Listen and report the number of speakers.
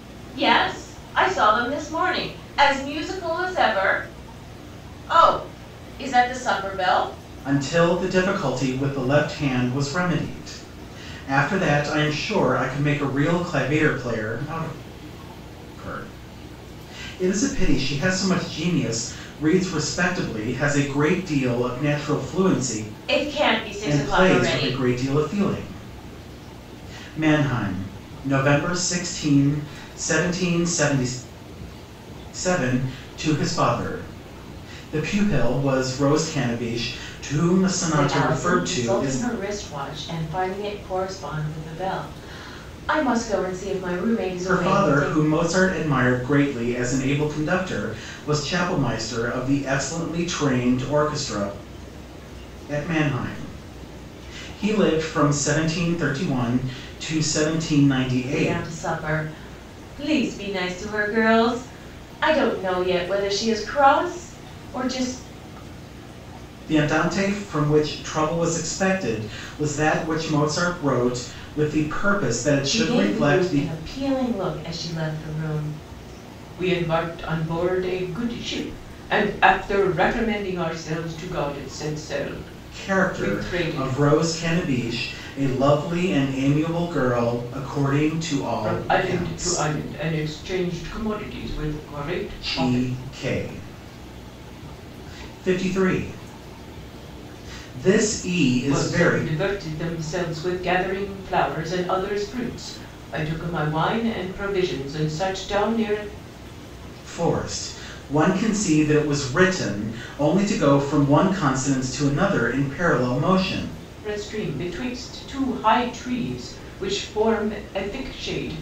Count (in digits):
2